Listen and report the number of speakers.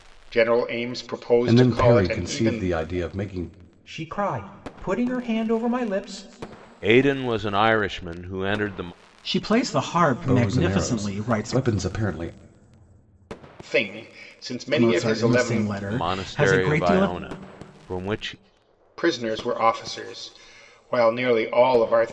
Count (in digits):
5